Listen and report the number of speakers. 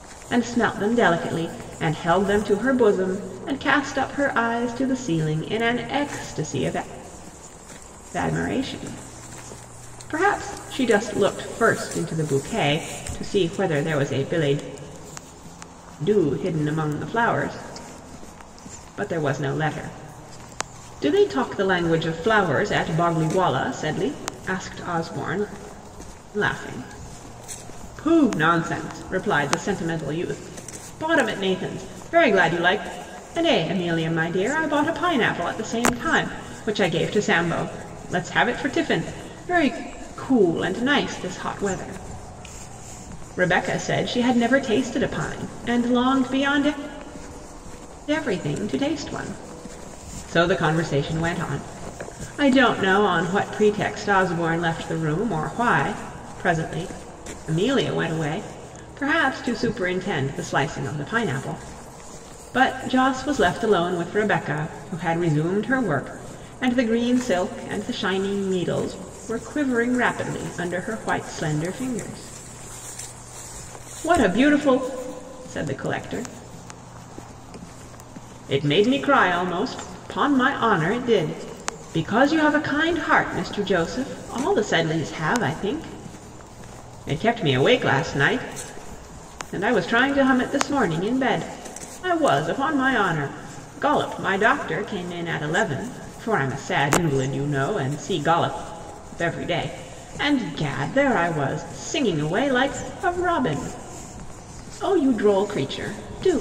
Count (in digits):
1